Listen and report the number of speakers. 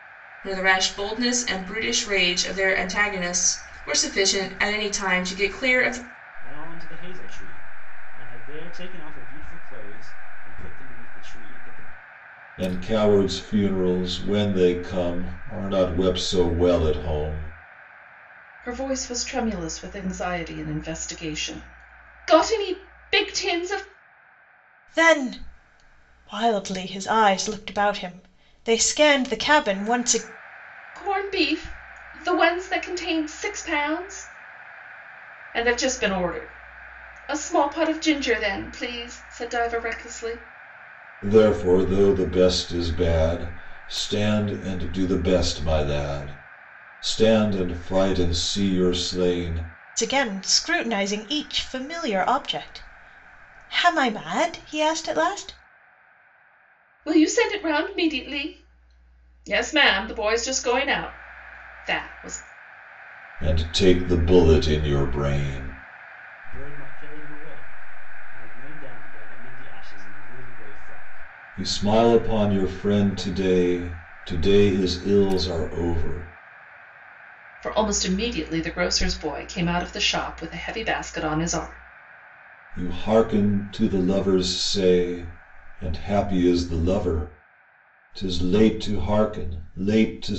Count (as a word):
five